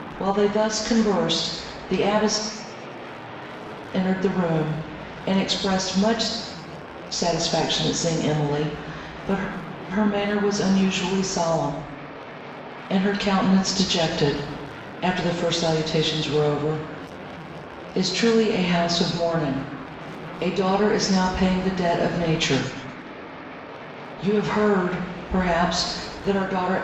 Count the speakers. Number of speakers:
one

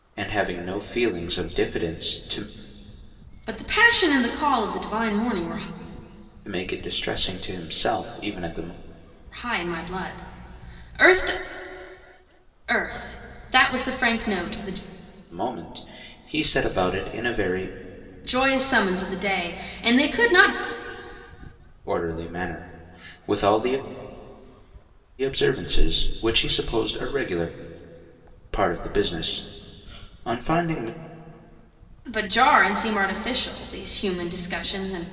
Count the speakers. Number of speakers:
two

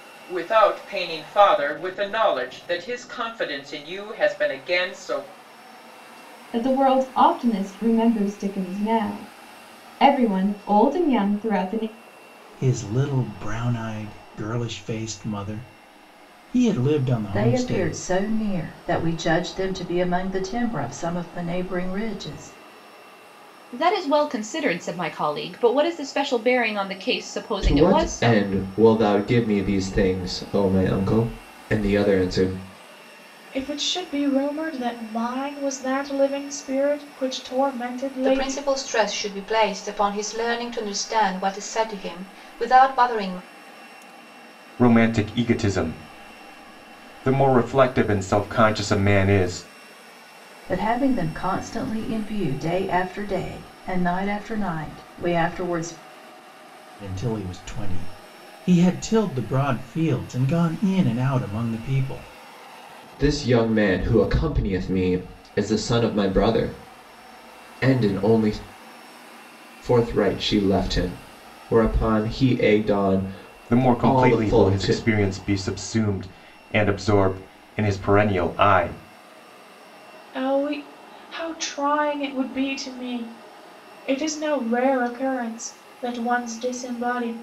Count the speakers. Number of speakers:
nine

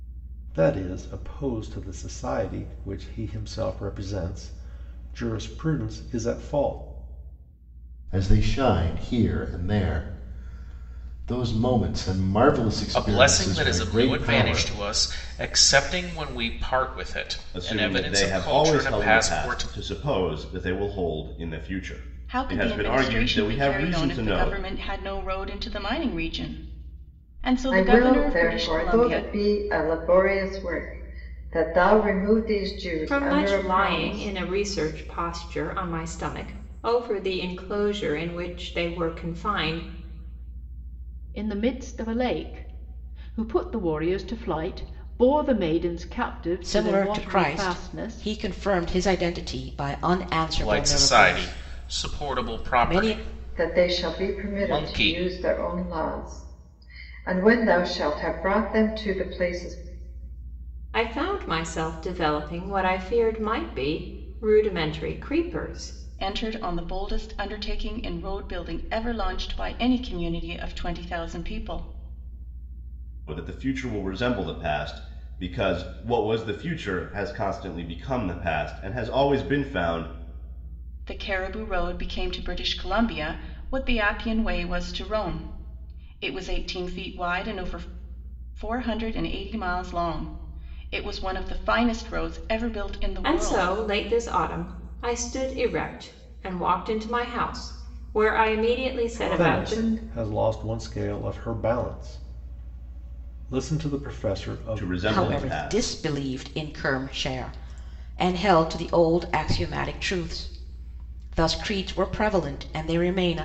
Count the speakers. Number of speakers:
nine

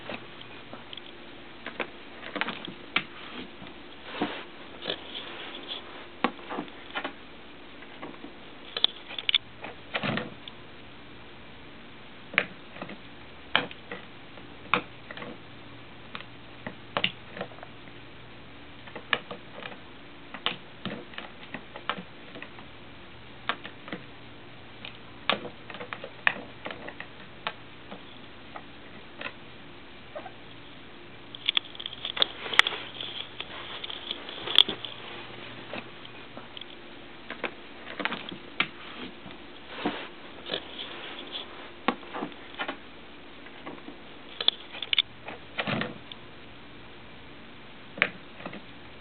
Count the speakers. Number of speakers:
zero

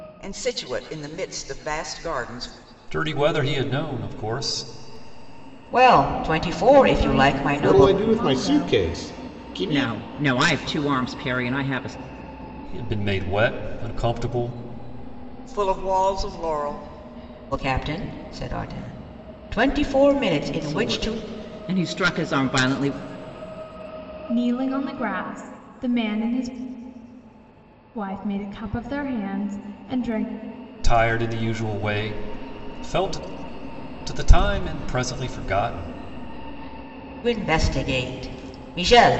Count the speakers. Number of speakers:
six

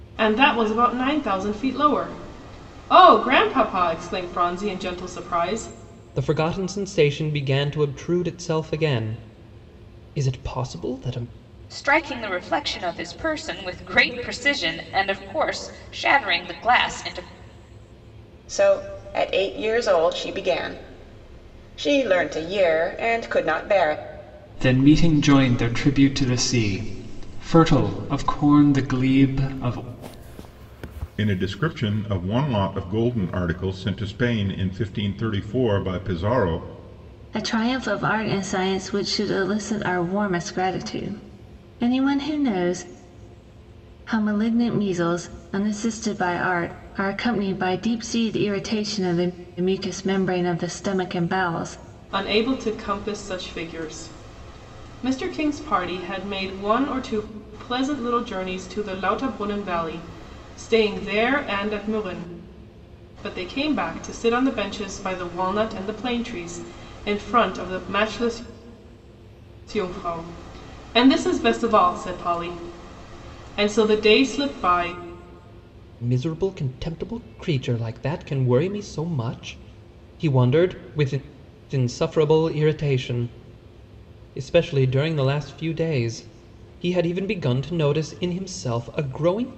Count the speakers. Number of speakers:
seven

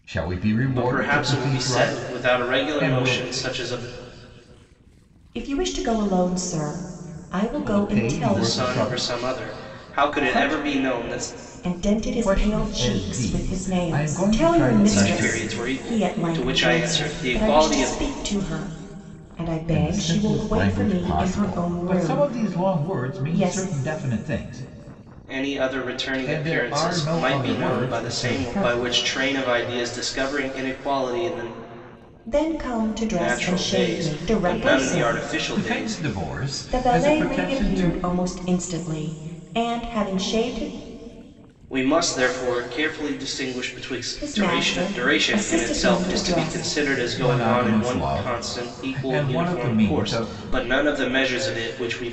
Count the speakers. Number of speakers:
three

